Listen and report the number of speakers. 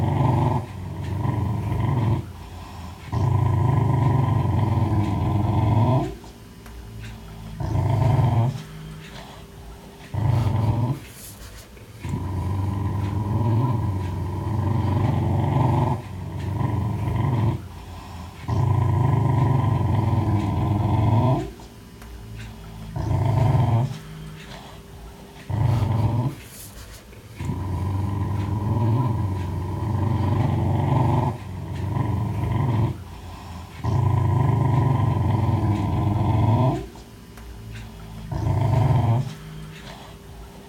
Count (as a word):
zero